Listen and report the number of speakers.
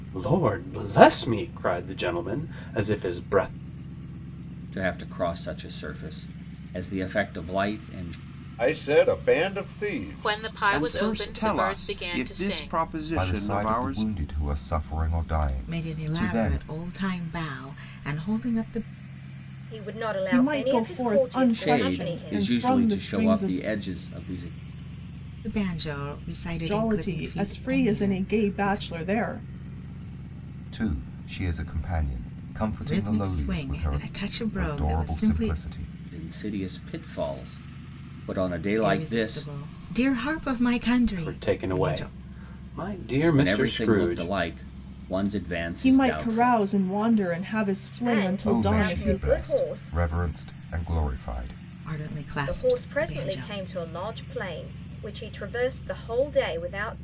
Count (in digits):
9